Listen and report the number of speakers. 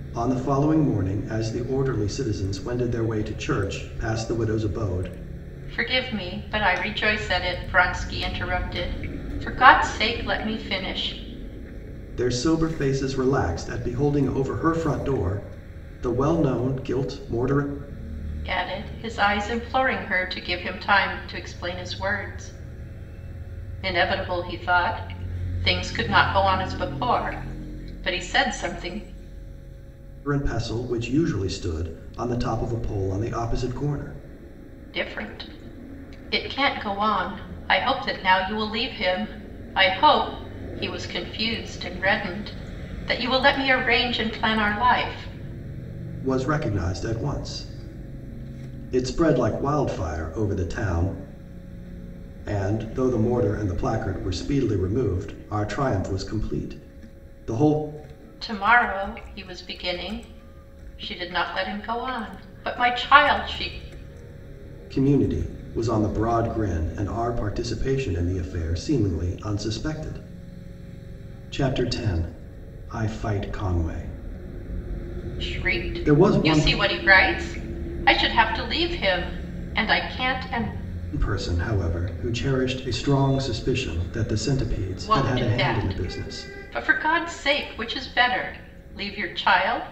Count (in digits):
2